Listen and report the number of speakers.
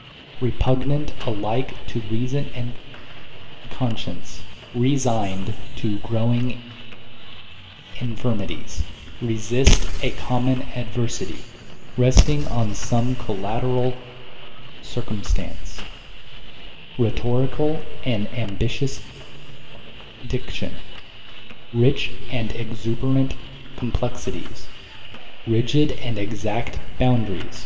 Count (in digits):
1